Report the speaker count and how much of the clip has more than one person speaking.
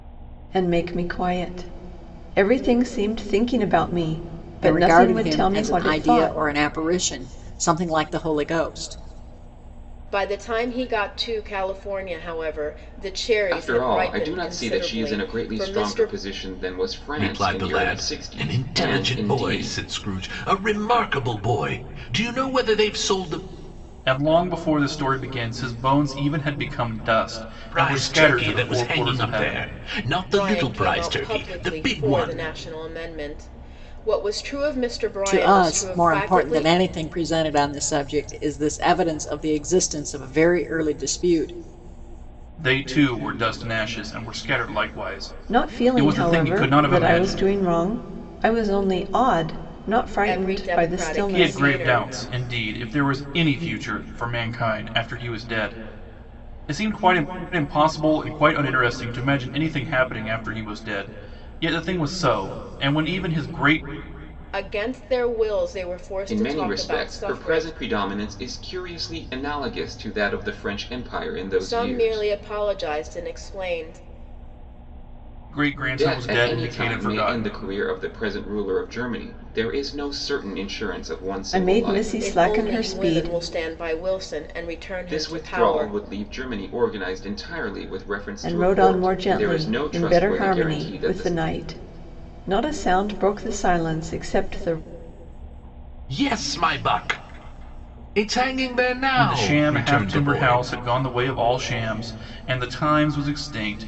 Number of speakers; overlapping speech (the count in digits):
6, about 27%